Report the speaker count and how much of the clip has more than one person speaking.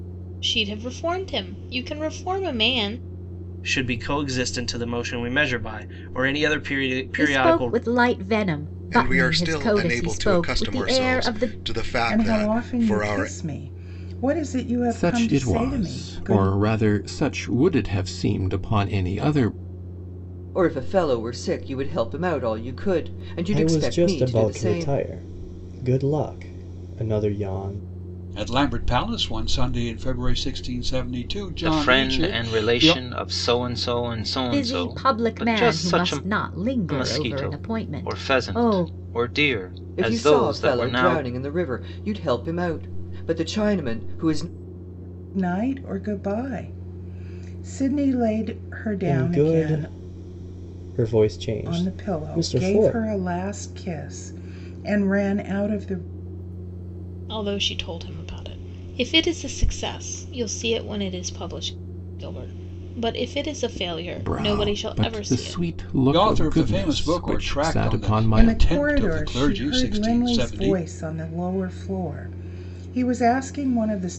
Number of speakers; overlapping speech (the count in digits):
10, about 31%